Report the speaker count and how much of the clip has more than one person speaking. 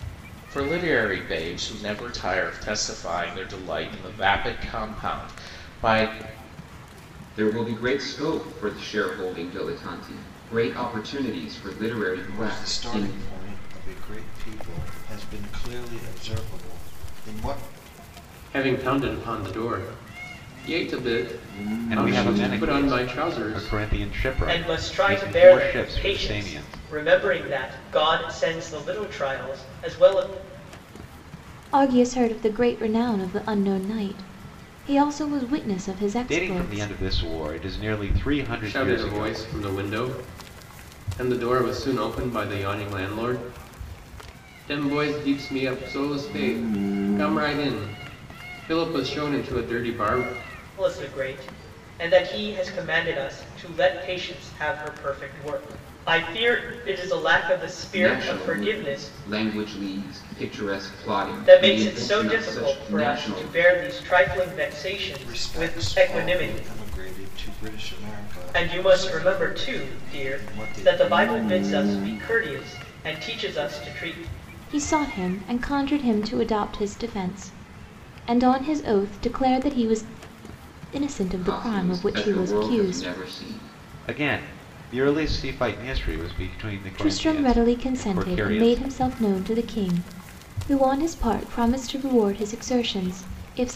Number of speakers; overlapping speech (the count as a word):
seven, about 19%